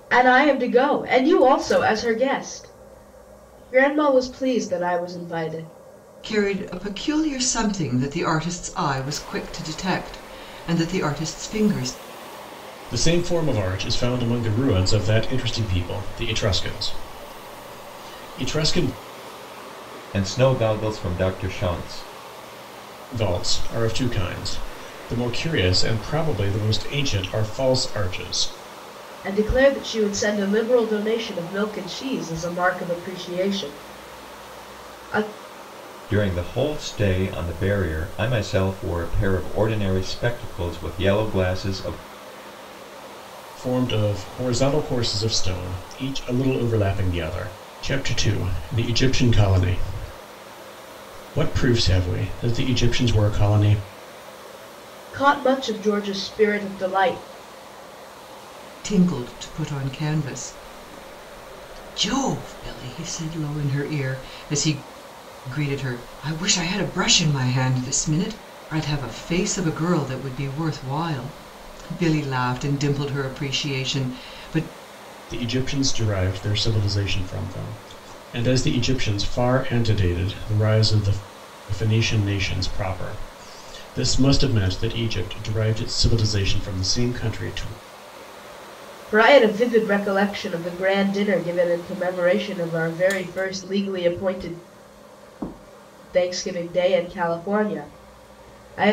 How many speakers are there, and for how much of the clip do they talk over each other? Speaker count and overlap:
4, no overlap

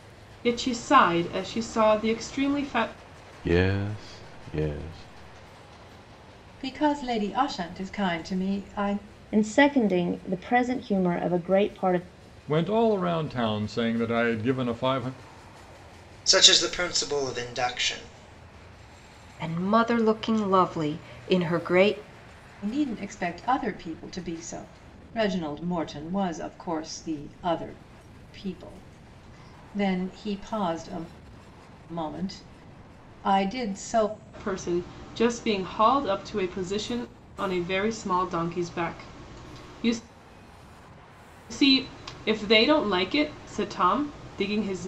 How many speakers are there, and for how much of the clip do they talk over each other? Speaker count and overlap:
7, no overlap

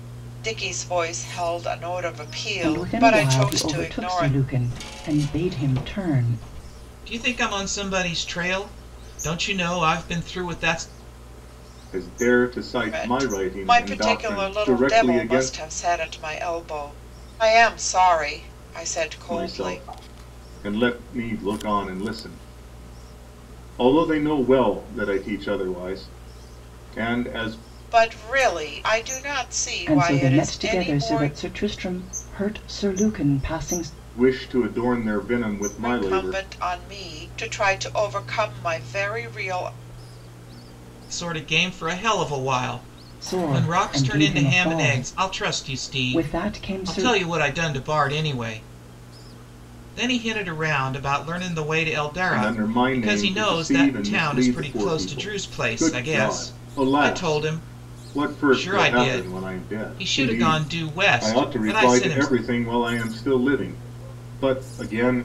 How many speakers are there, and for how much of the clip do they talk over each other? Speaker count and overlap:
4, about 31%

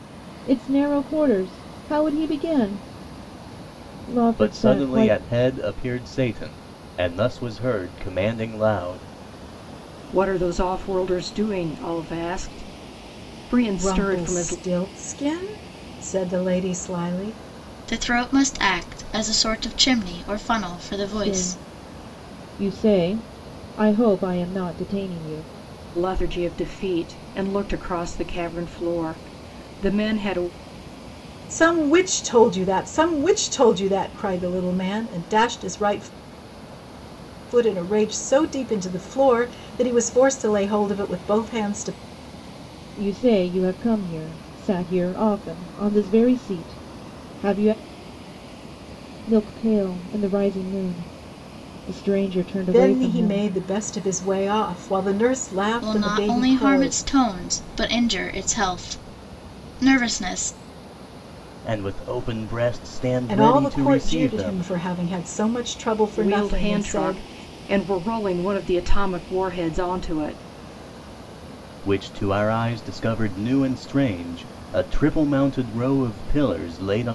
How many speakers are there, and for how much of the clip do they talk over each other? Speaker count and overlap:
5, about 9%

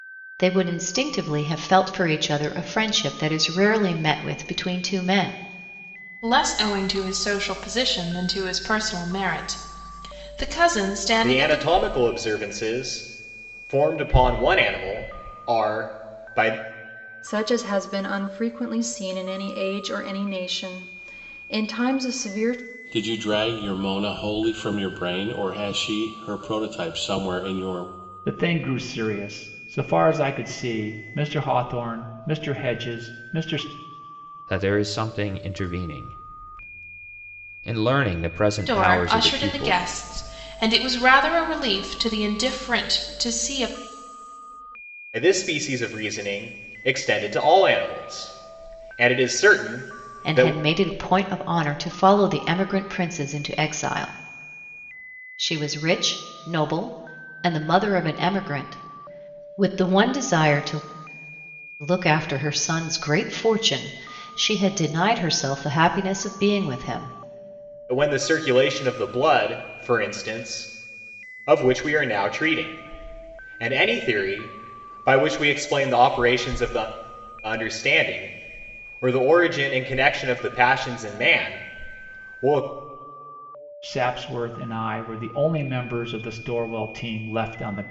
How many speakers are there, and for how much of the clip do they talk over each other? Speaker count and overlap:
7, about 2%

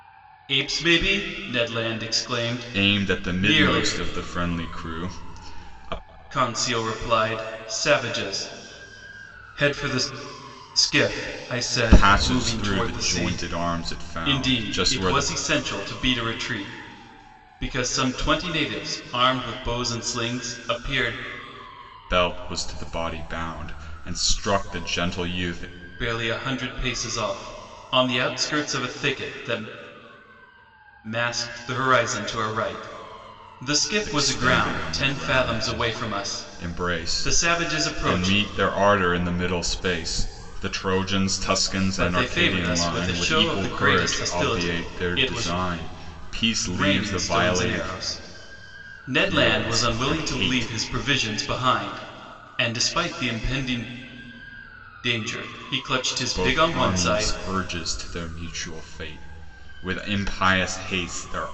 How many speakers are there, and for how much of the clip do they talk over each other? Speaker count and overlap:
2, about 24%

